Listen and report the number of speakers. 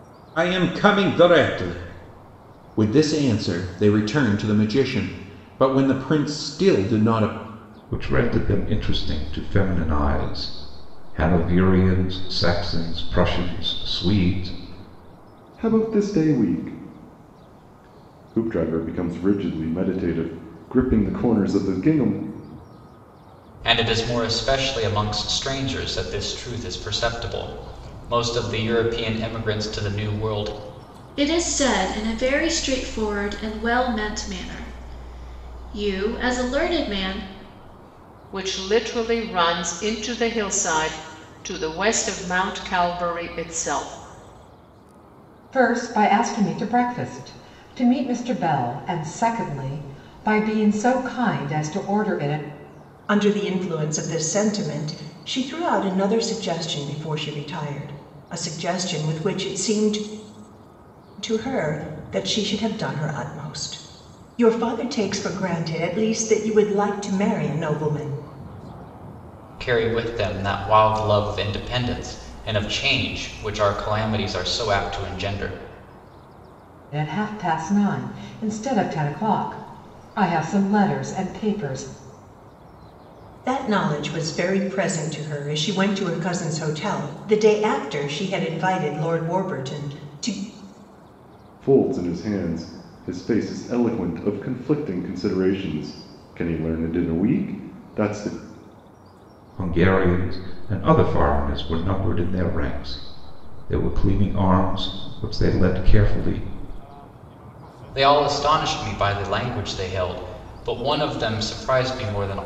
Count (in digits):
8